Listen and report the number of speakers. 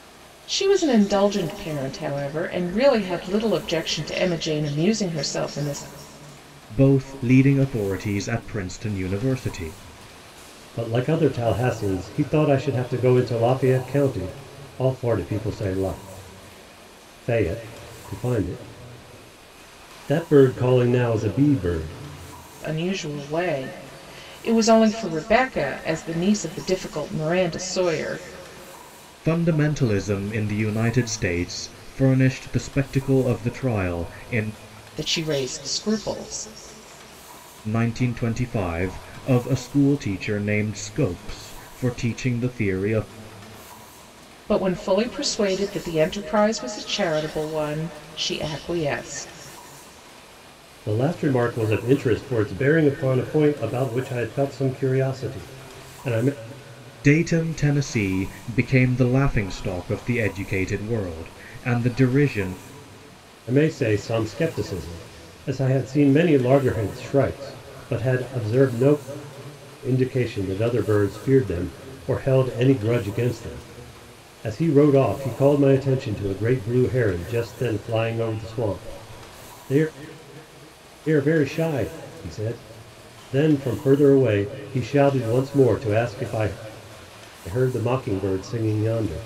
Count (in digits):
3